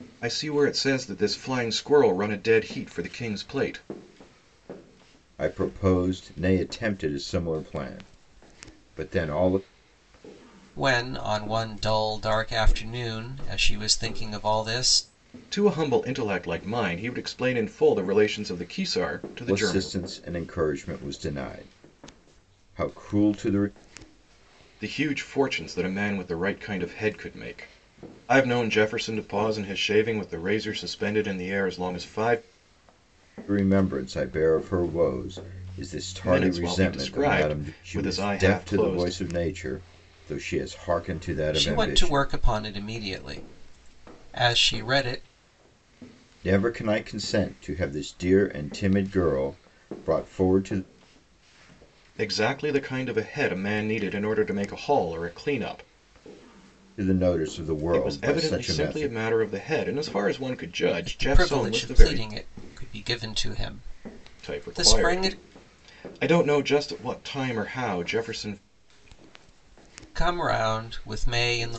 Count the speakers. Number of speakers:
3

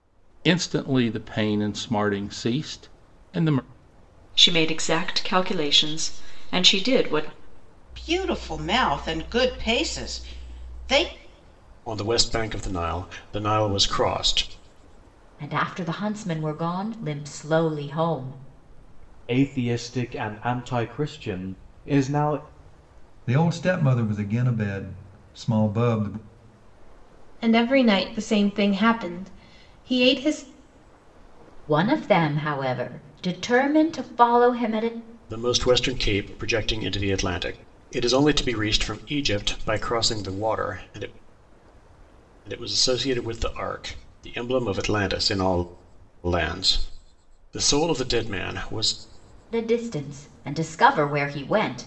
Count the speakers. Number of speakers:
8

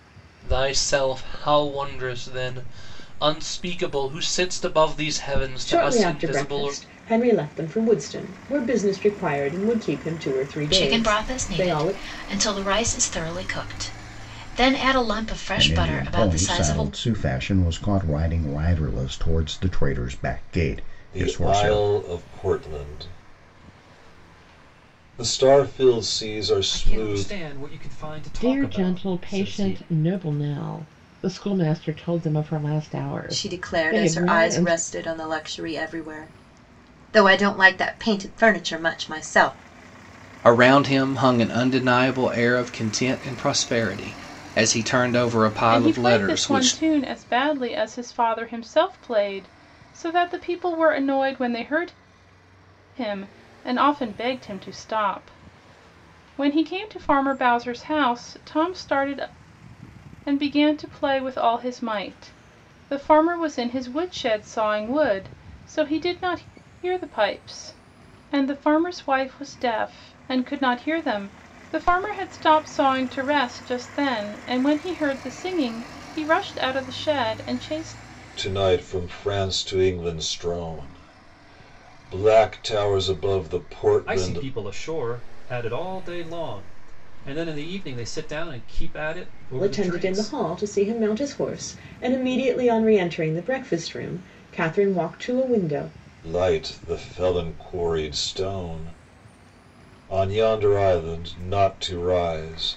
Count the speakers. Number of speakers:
10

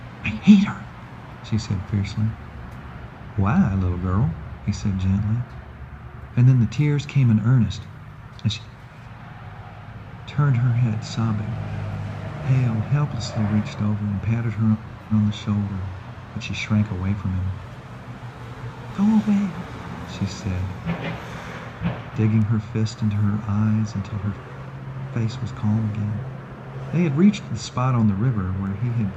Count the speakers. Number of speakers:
1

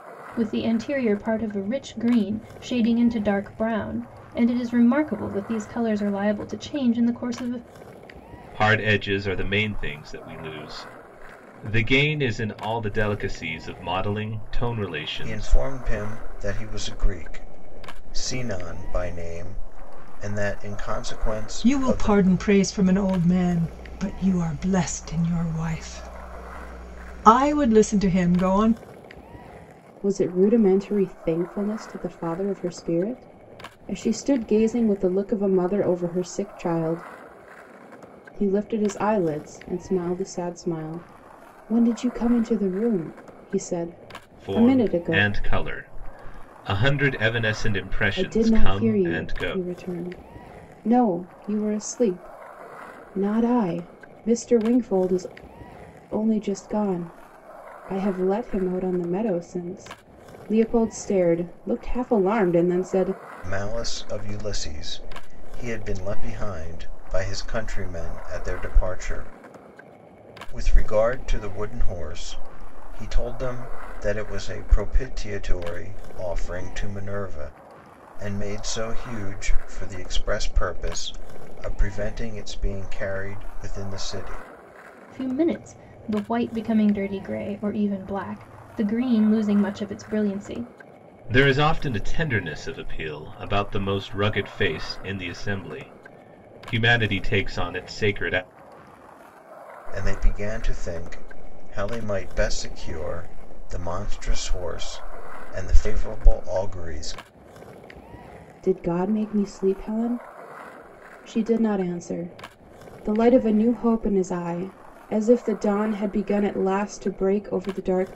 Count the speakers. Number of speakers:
5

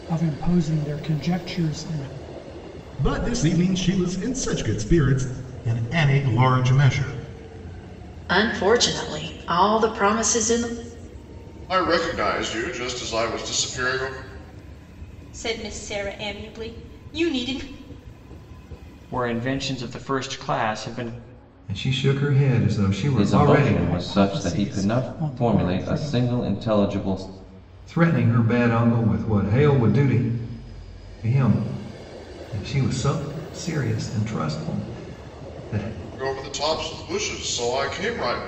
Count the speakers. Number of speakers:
9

